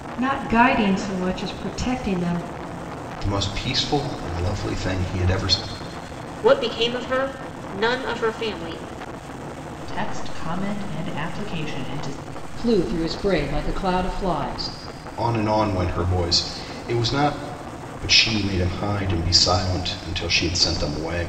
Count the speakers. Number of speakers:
5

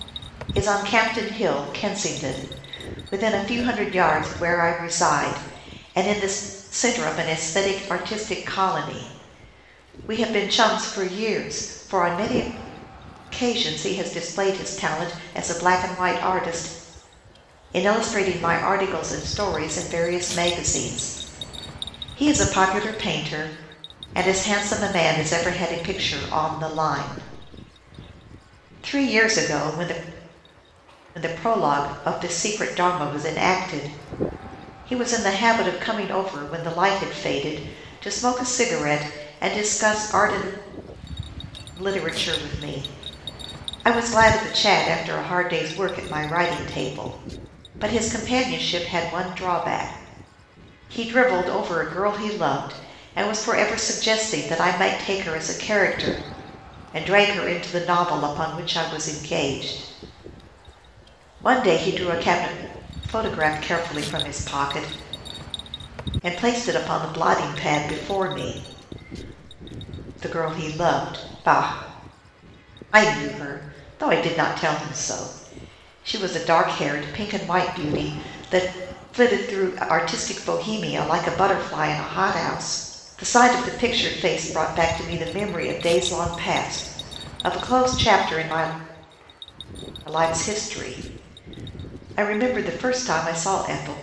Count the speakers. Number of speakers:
1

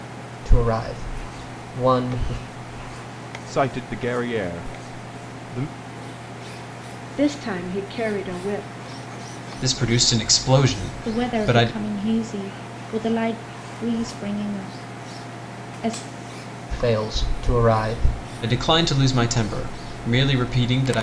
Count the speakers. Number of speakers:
5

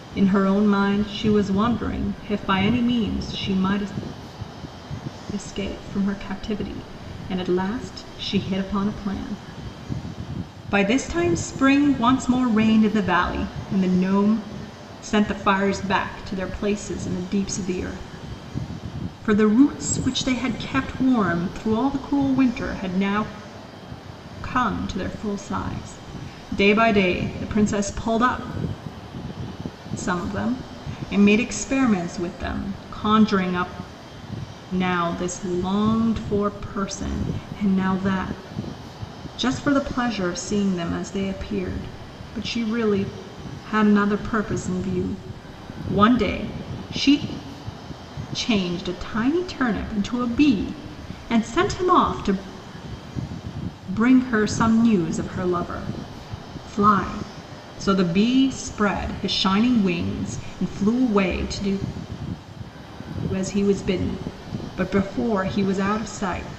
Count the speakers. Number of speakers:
1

